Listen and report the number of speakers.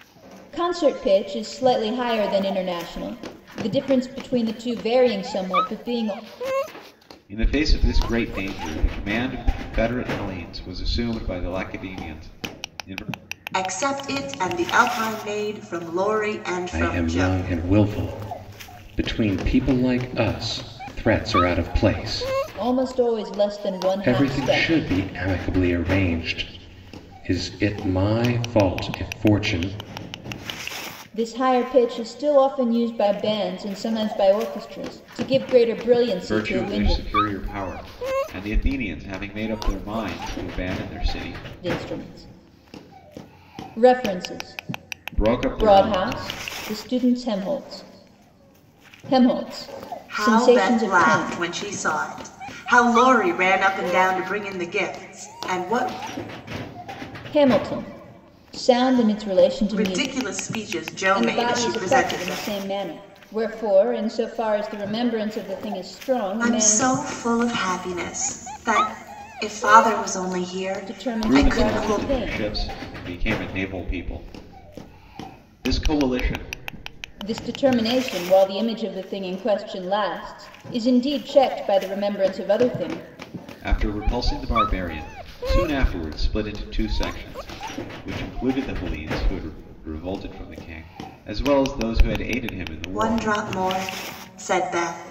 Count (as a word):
four